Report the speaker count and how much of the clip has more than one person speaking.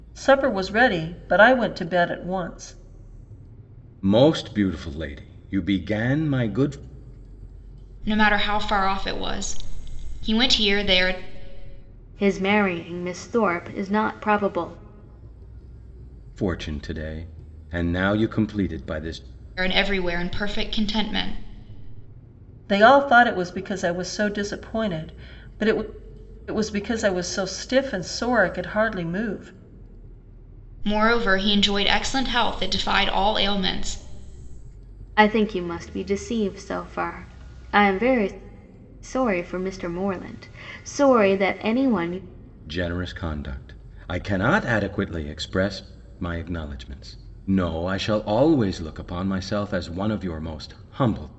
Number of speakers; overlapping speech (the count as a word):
four, no overlap